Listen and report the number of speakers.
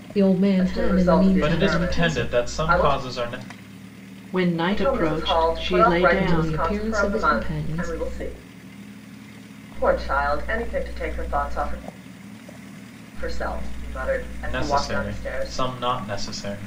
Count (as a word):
four